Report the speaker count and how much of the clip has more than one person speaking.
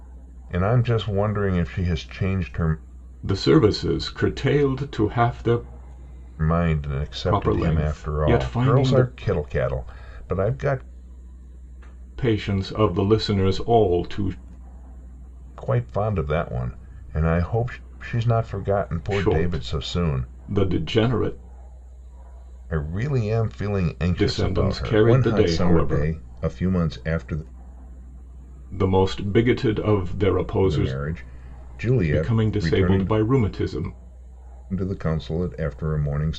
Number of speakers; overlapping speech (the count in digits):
2, about 18%